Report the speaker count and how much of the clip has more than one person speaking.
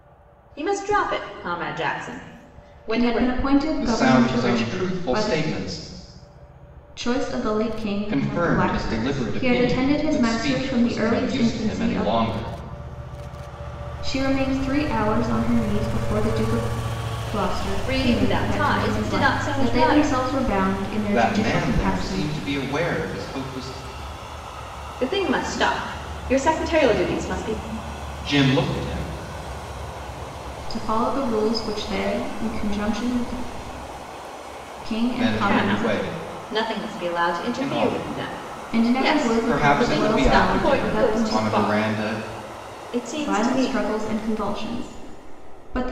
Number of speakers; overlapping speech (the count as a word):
three, about 36%